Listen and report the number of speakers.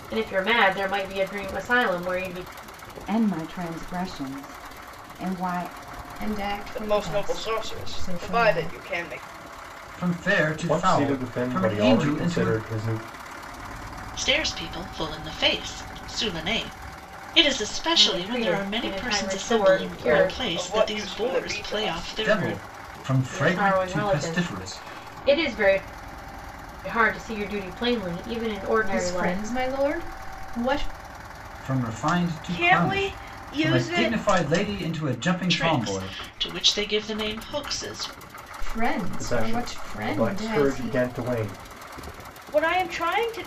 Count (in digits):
7